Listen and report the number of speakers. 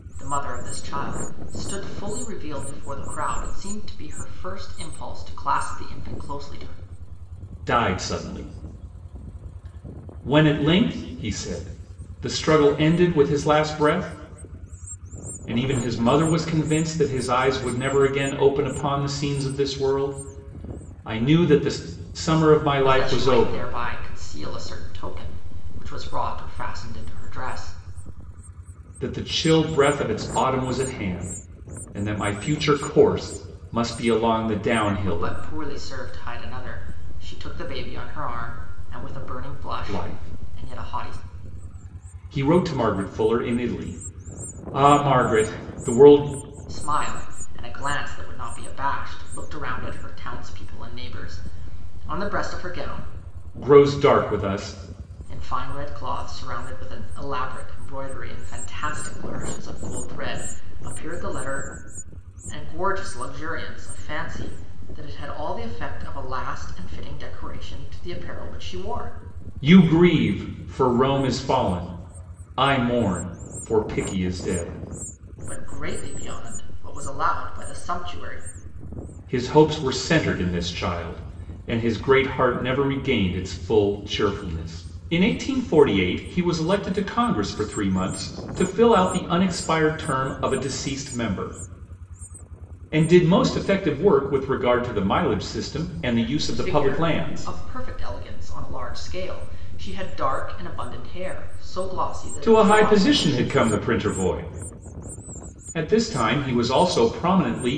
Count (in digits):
2